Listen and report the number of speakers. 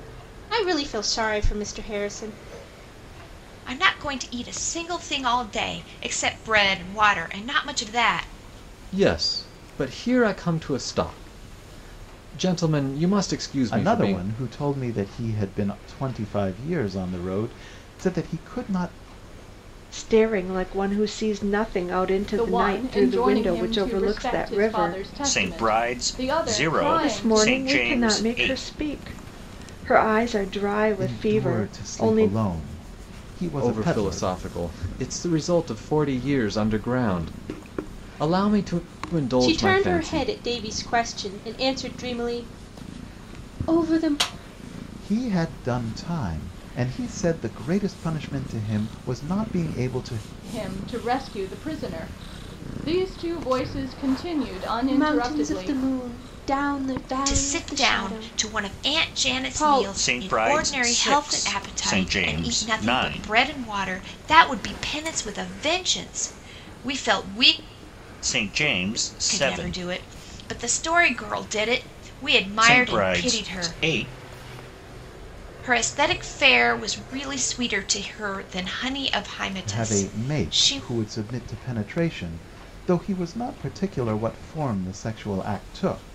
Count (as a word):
seven